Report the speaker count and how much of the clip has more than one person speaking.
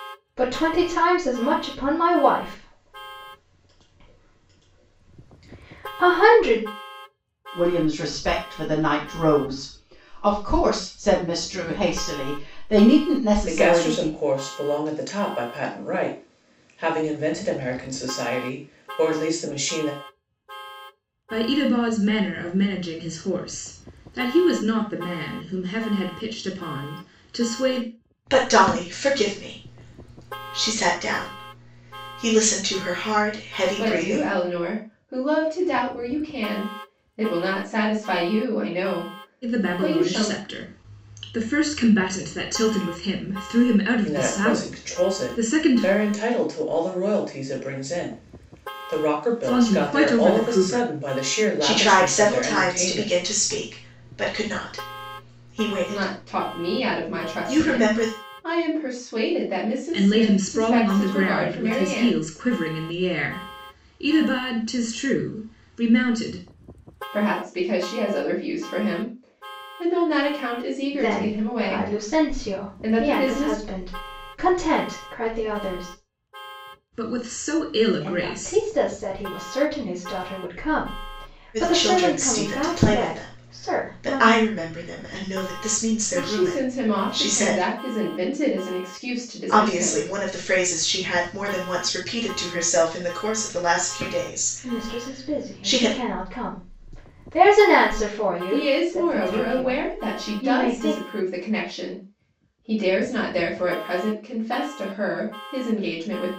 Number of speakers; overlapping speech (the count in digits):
6, about 23%